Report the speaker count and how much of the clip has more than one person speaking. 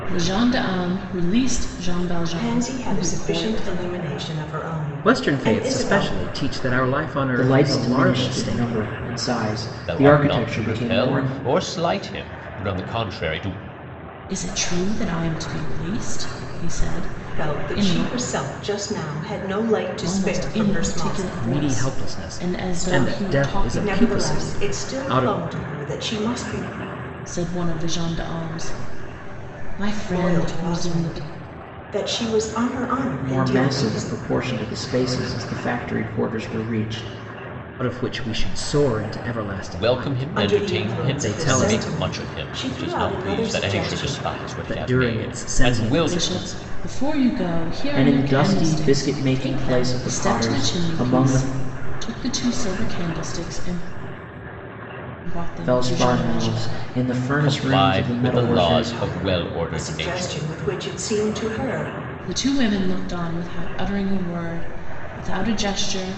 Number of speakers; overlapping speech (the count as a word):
five, about 43%